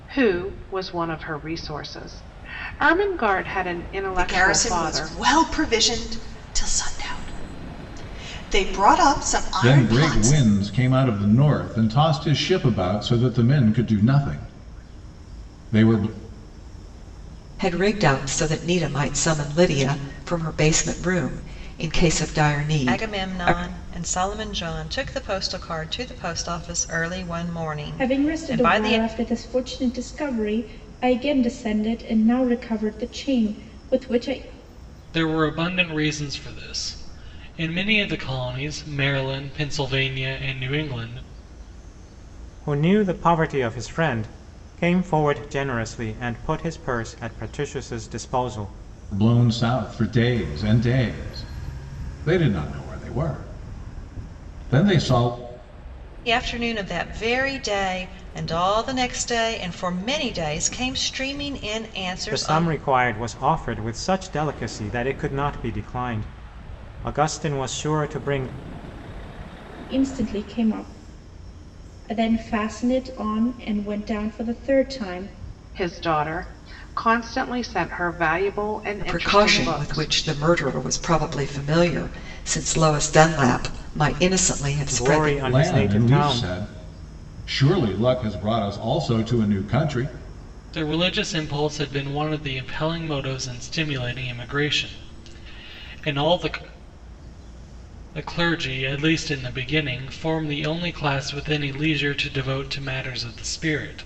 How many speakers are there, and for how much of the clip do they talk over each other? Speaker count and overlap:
8, about 7%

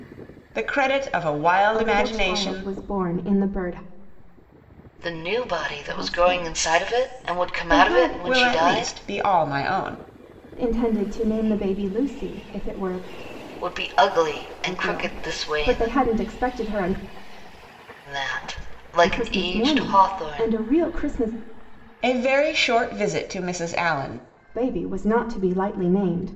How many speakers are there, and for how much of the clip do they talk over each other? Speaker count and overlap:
3, about 26%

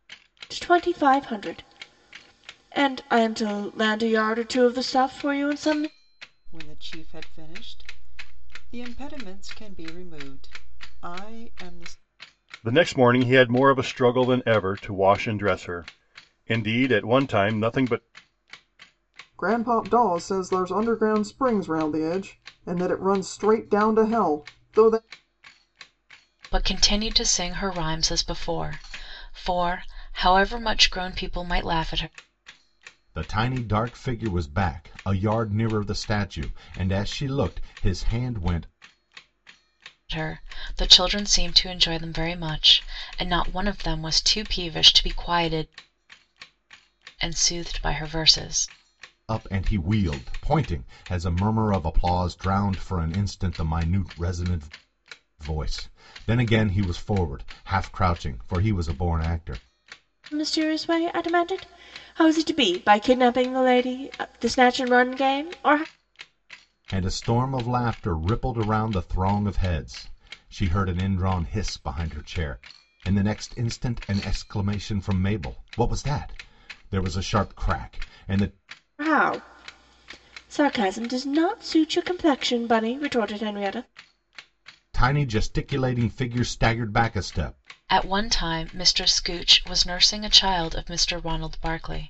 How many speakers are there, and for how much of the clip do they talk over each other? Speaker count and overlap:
6, no overlap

